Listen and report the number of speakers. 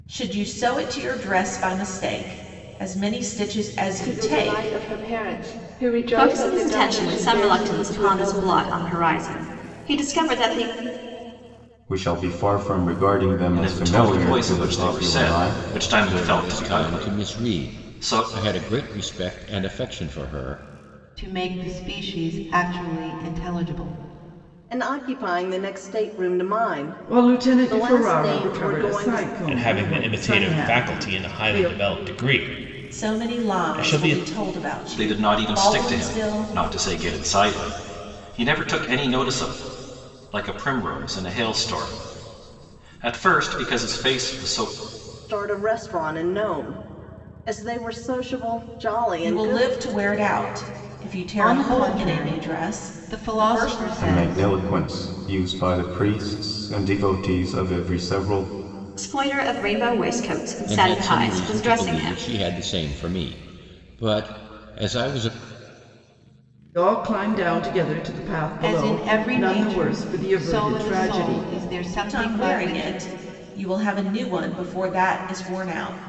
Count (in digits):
10